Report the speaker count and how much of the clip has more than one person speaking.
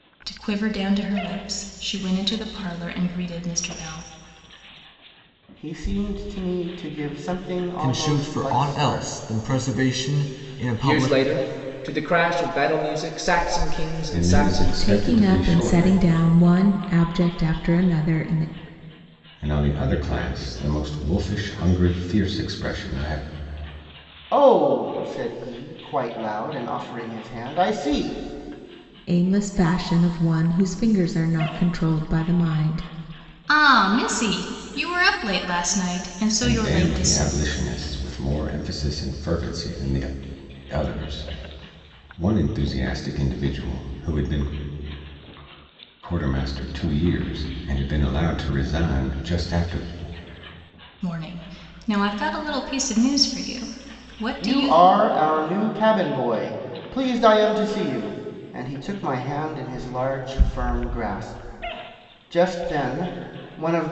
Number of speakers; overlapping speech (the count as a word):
six, about 8%